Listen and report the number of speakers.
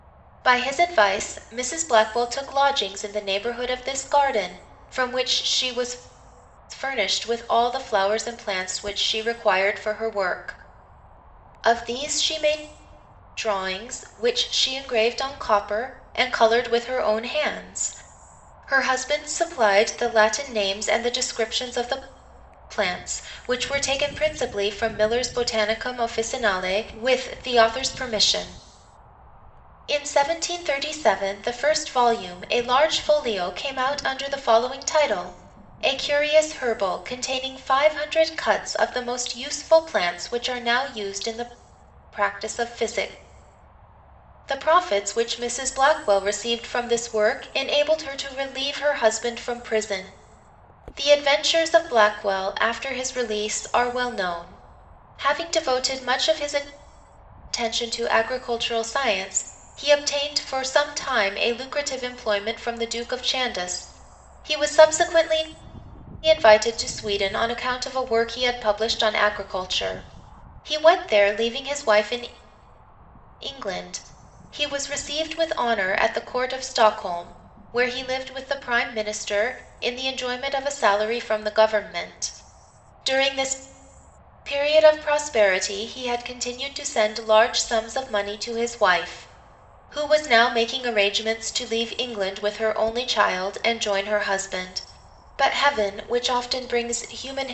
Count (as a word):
one